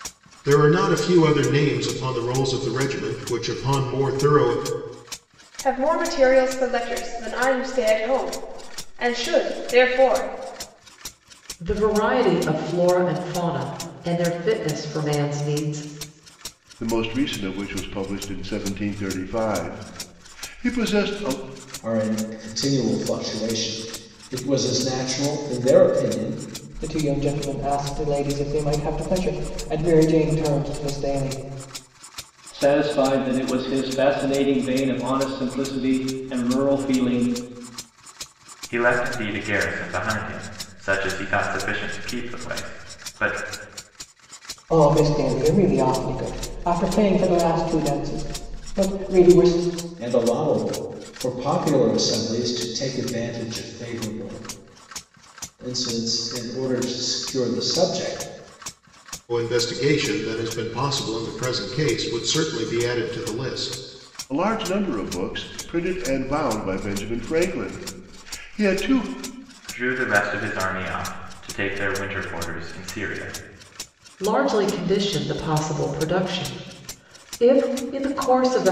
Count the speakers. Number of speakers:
8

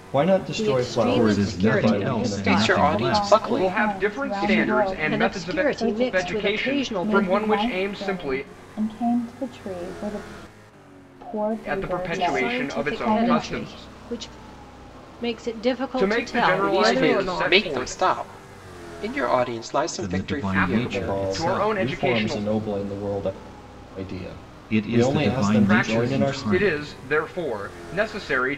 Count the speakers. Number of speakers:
6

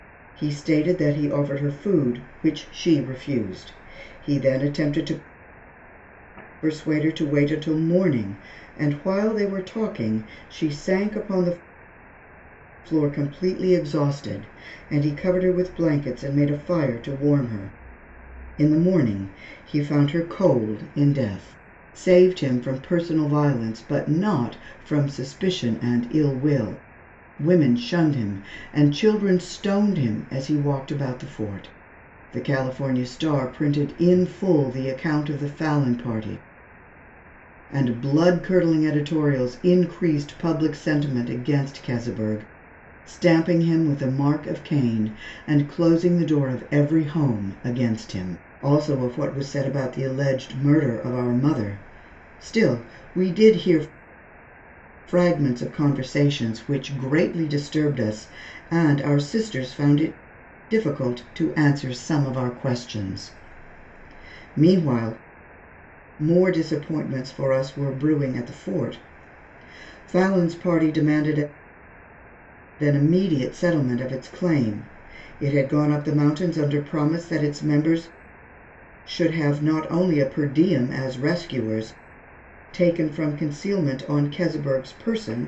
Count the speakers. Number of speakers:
1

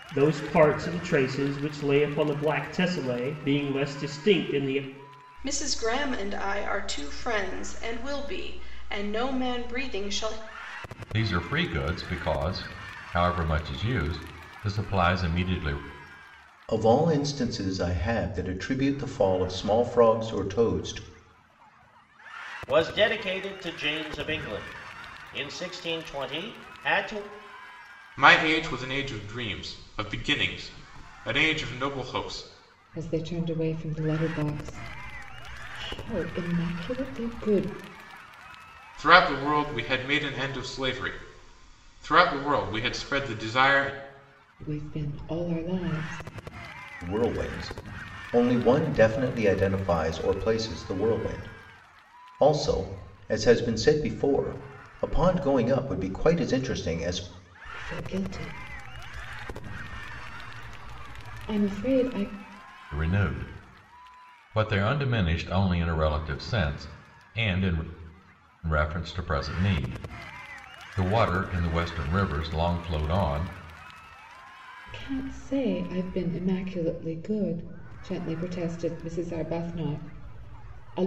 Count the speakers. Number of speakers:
7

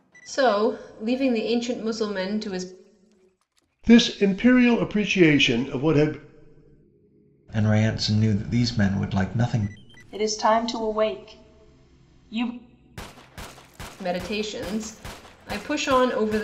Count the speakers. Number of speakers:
4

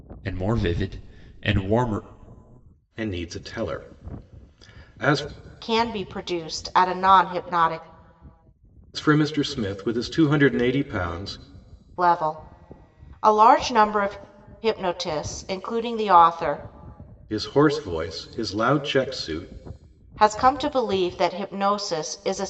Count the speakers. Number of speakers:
3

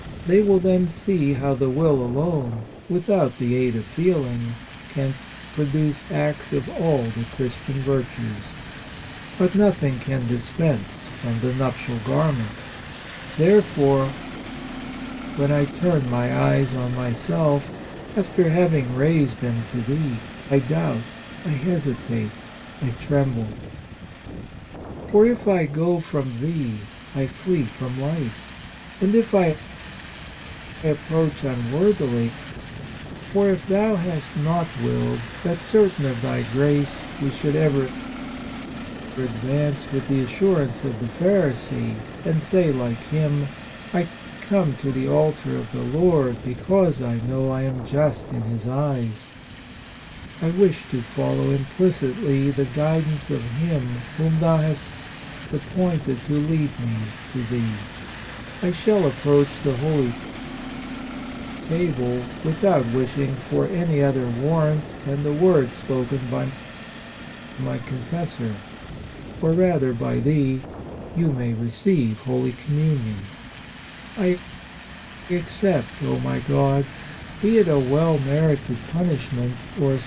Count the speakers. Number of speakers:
1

